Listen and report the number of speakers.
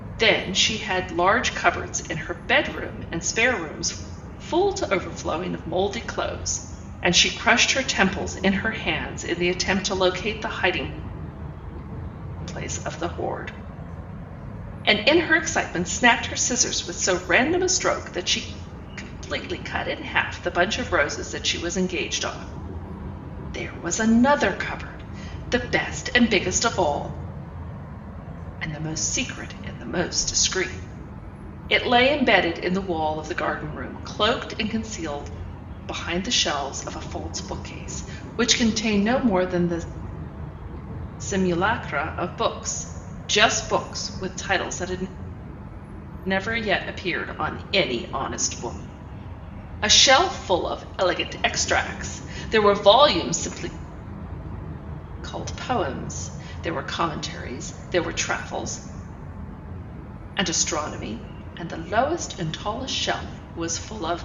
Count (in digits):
1